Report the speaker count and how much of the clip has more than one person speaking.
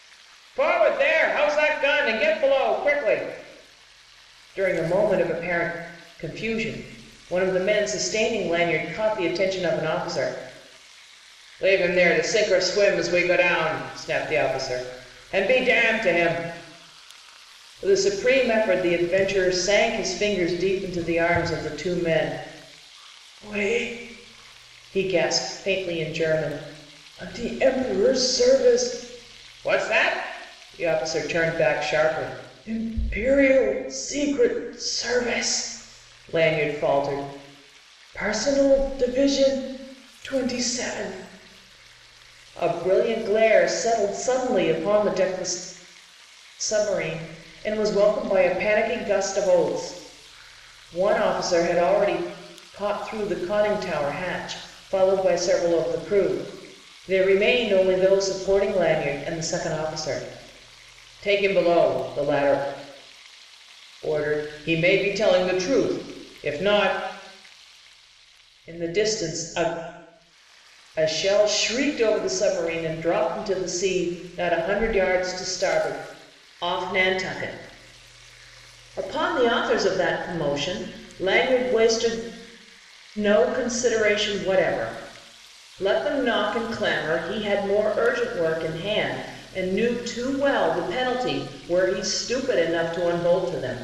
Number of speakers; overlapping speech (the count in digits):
1, no overlap